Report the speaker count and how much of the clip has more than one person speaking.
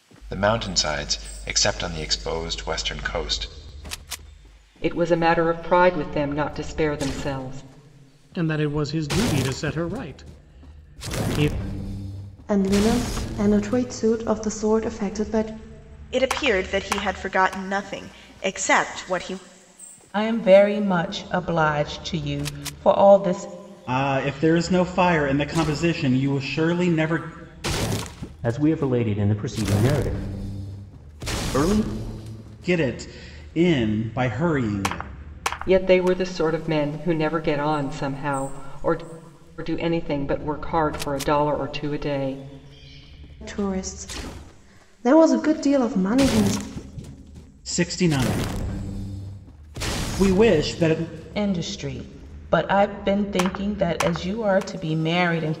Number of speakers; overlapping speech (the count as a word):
eight, no overlap